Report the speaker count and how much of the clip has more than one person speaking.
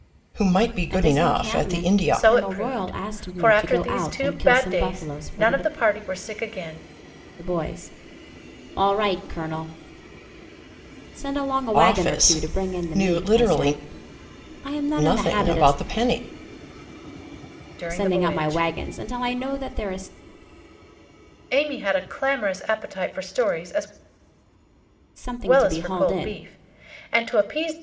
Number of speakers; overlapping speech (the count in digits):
3, about 33%